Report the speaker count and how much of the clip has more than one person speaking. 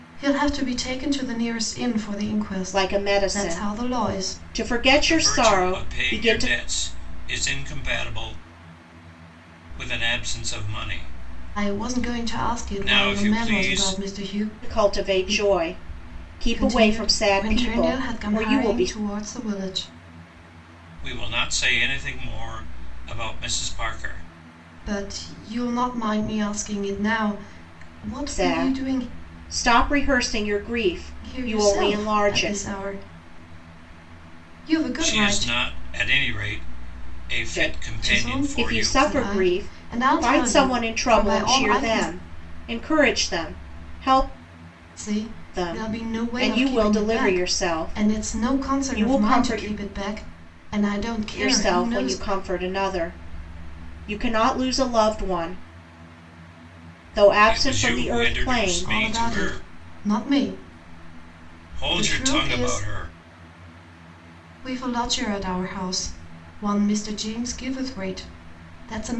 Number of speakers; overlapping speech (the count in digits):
3, about 34%